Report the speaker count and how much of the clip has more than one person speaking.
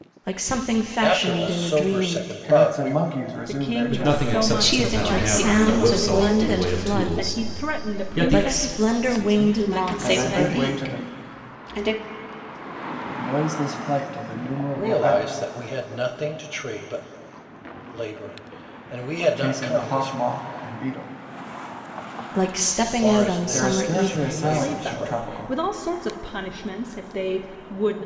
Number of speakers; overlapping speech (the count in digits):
6, about 49%